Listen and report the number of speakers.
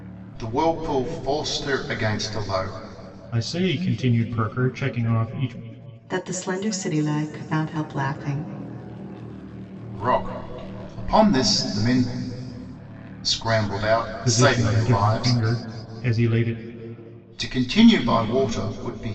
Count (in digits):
3